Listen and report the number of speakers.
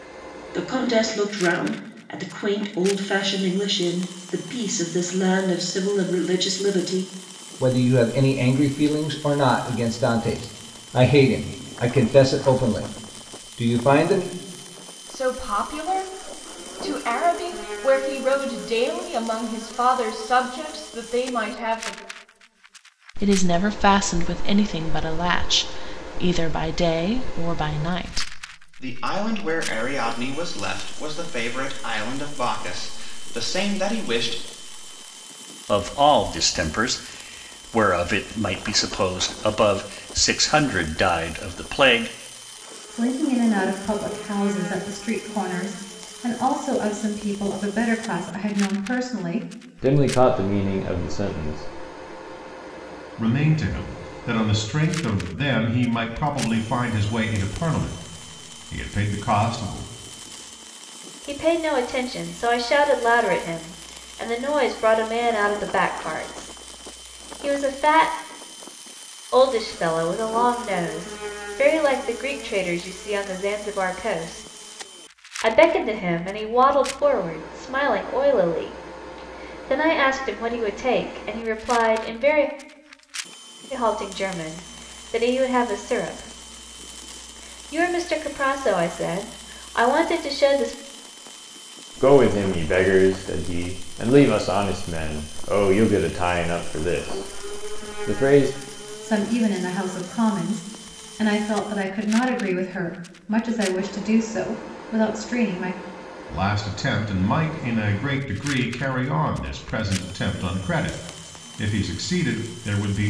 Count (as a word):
ten